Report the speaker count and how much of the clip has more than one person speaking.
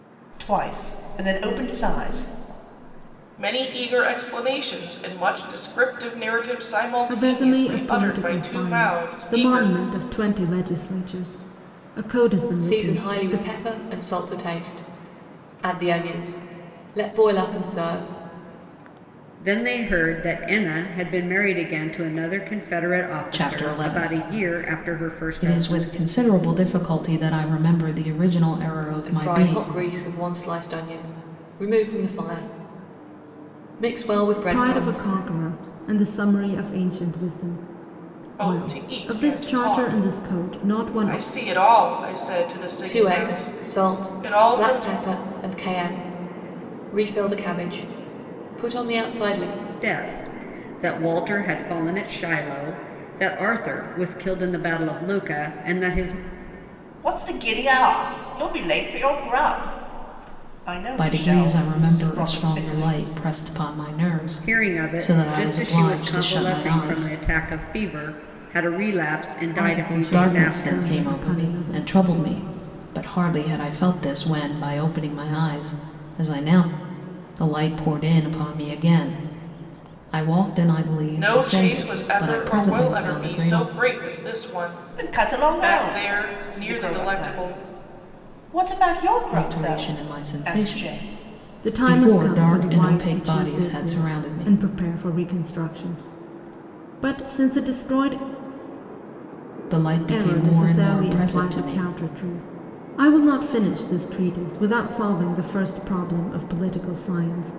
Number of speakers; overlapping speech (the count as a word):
six, about 29%